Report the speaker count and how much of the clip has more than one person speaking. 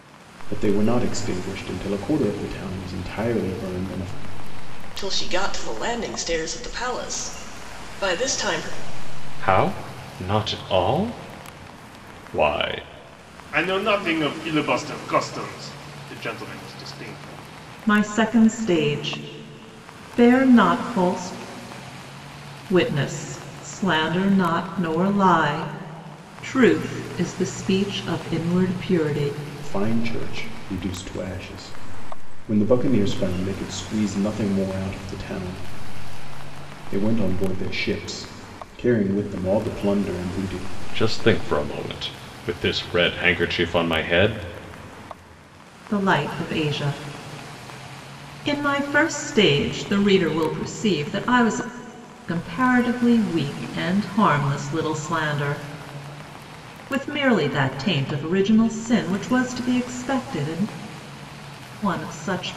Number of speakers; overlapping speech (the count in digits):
5, no overlap